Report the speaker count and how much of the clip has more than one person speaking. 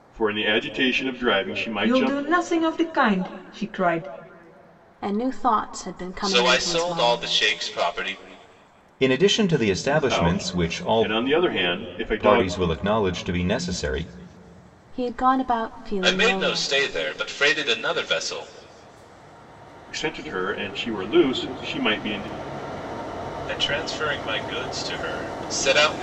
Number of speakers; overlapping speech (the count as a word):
five, about 14%